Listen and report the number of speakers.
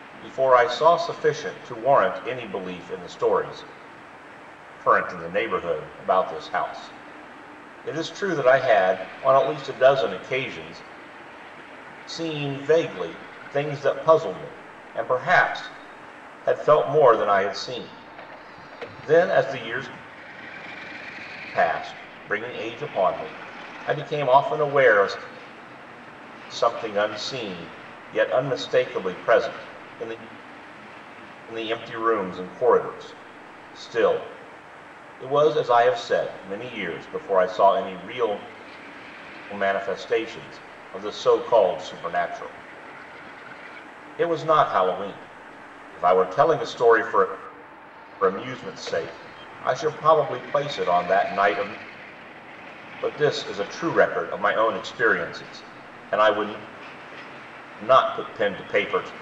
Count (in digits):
1